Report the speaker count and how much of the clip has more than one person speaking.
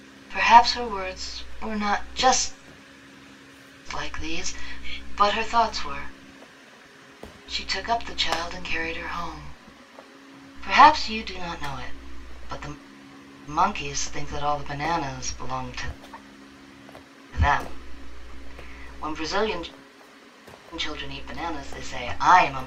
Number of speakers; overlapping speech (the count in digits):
1, no overlap